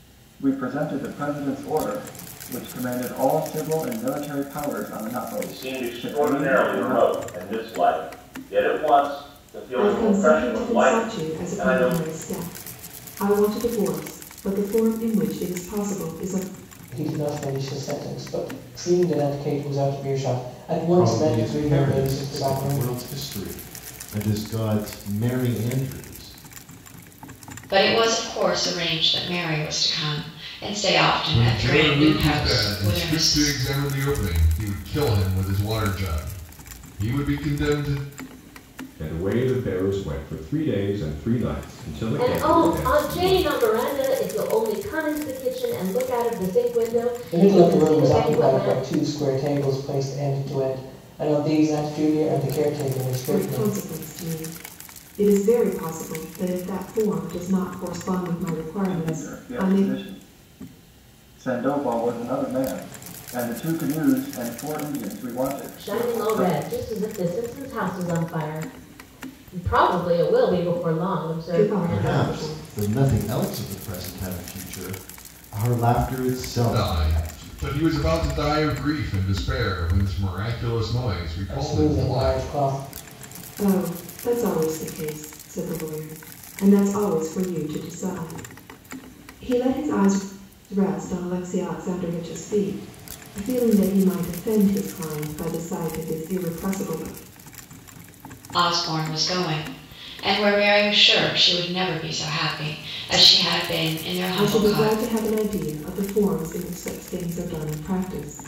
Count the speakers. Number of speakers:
nine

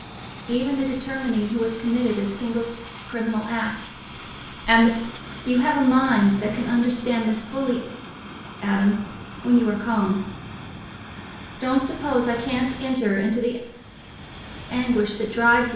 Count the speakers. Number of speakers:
one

